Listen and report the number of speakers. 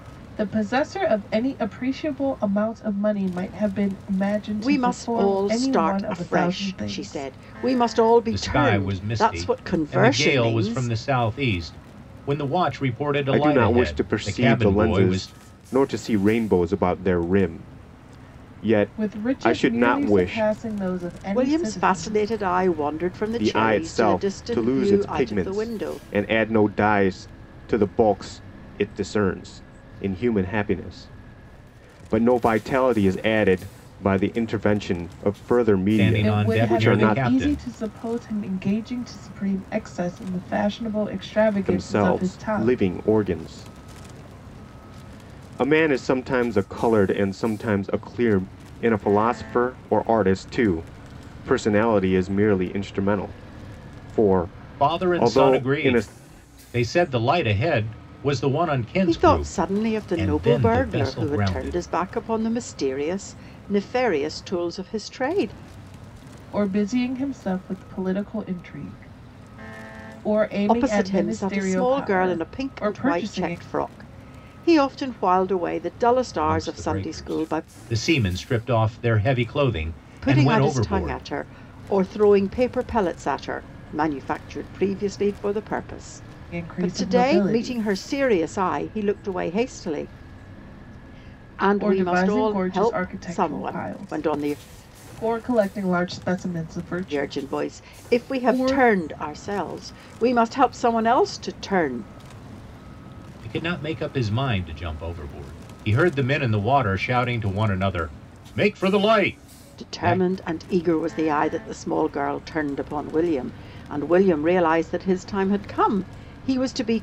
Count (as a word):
four